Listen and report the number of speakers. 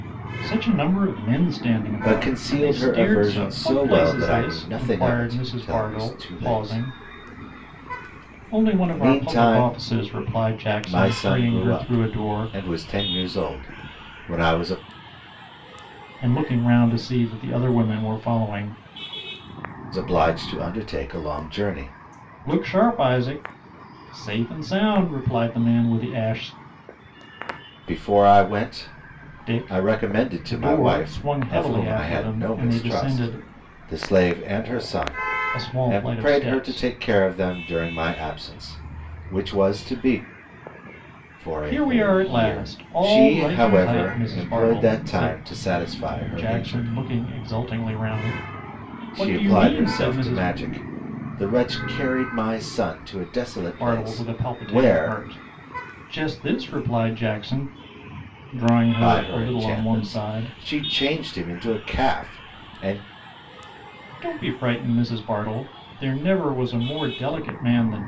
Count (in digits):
2